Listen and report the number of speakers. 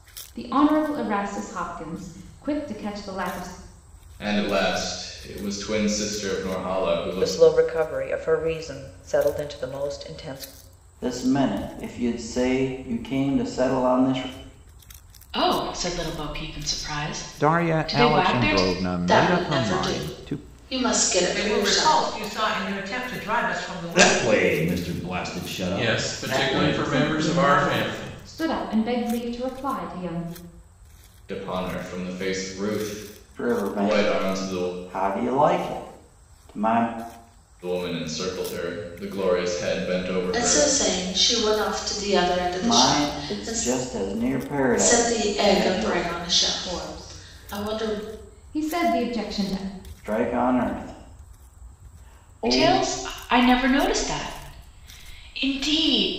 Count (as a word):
ten